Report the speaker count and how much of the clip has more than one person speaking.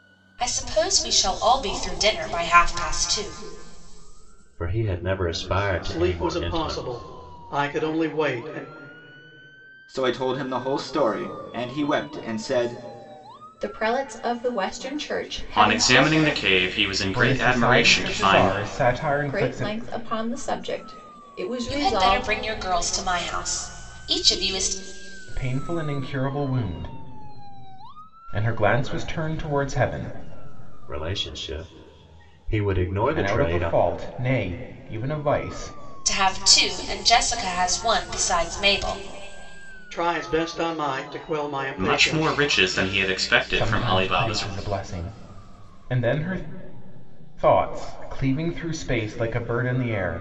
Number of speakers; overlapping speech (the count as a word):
seven, about 15%